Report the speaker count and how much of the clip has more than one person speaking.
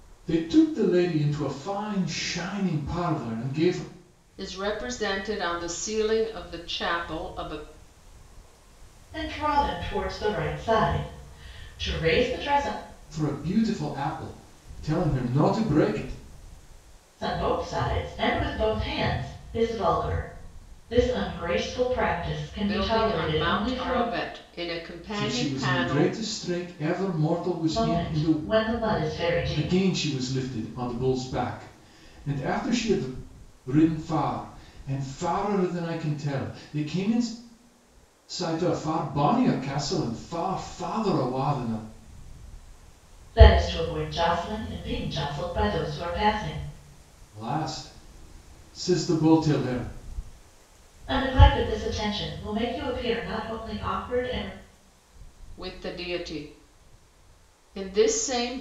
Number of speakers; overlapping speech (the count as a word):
three, about 6%